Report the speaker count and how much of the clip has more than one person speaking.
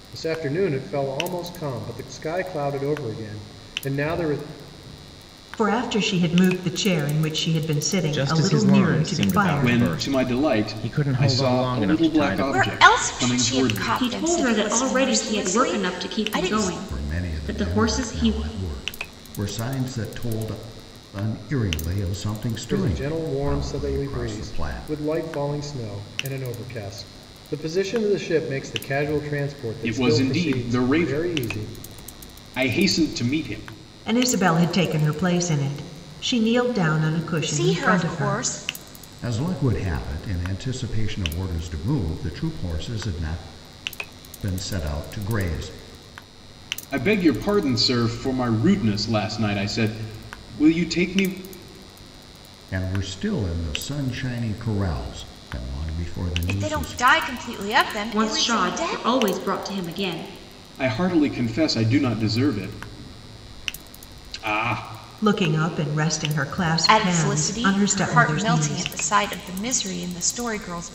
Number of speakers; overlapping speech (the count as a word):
seven, about 27%